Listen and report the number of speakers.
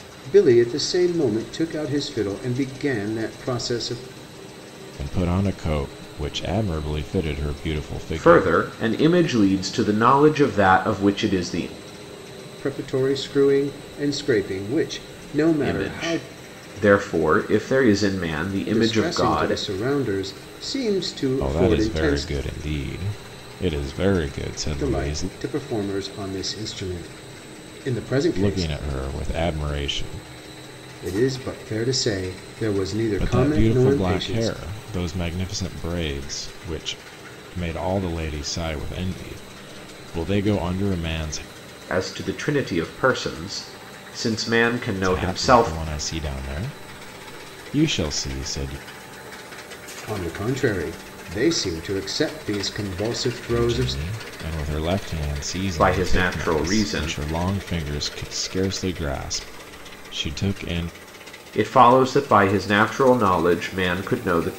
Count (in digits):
3